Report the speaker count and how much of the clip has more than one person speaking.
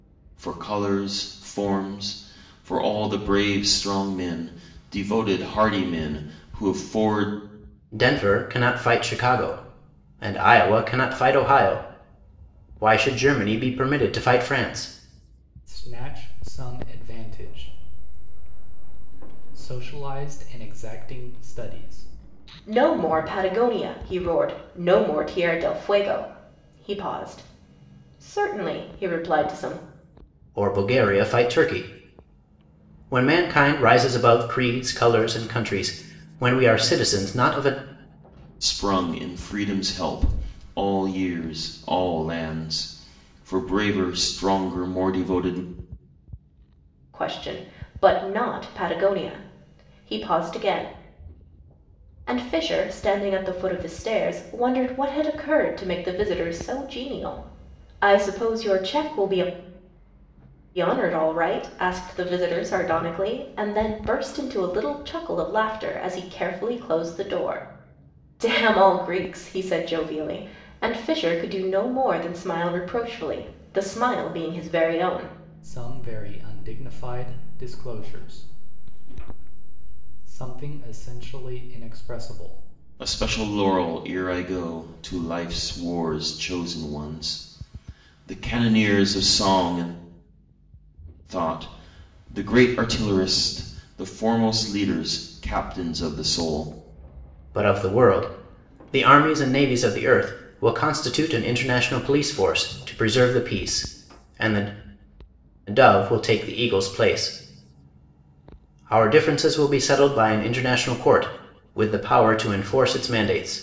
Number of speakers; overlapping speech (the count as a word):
four, no overlap